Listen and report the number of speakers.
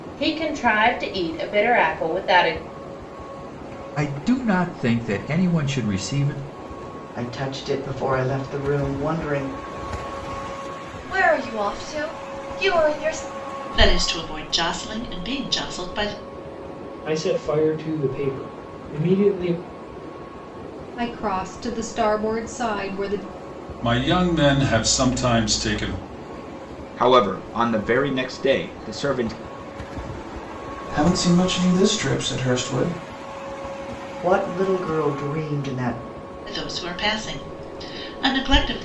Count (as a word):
ten